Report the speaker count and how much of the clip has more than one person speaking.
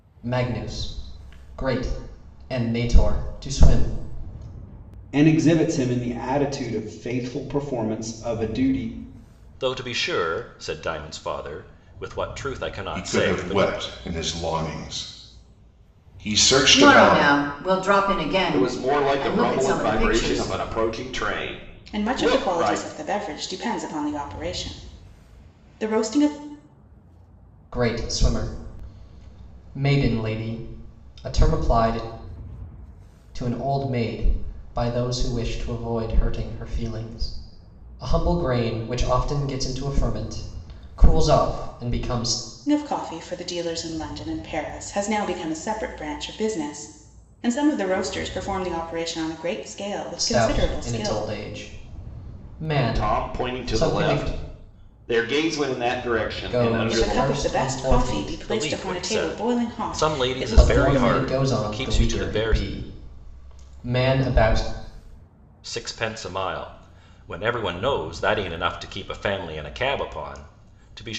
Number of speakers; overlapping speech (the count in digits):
7, about 19%